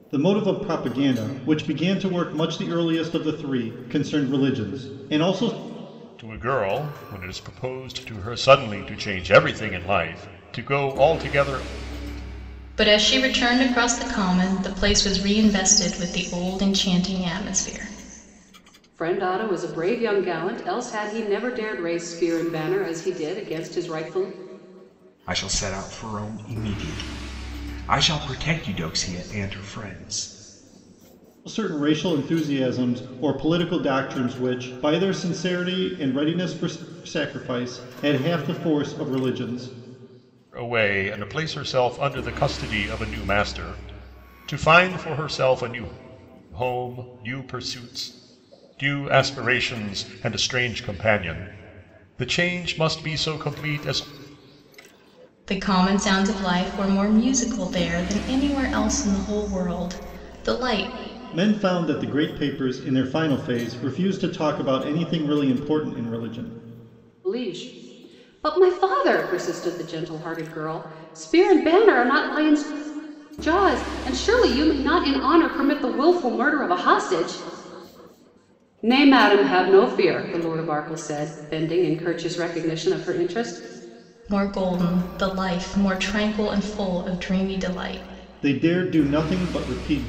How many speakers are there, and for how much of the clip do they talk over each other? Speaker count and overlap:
five, no overlap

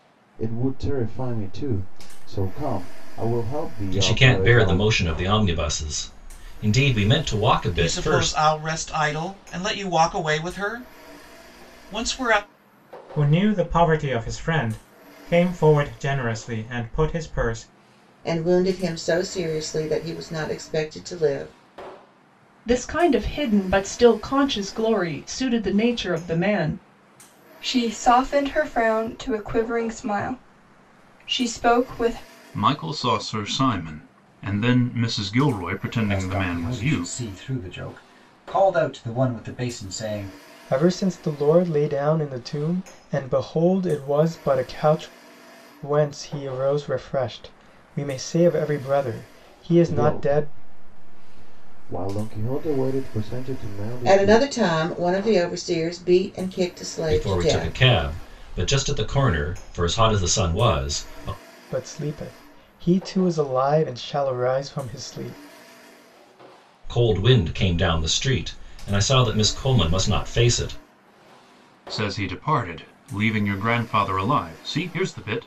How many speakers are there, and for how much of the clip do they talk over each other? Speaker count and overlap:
ten, about 6%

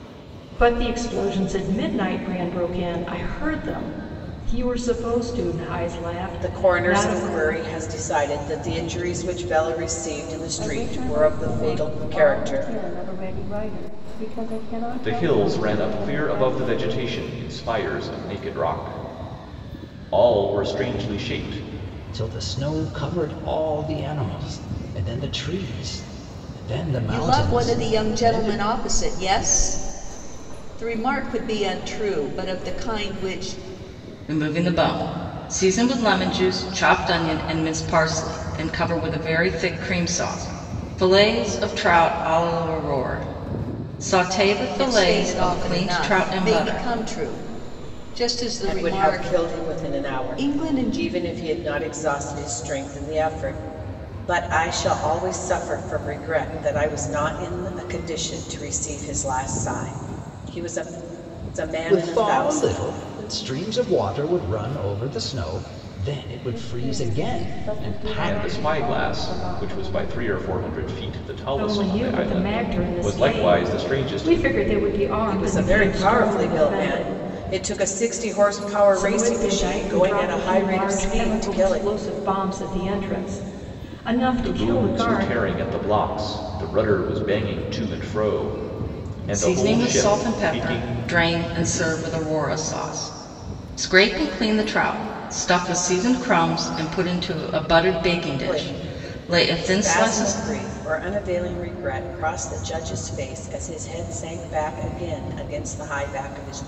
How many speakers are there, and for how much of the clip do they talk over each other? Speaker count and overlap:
seven, about 27%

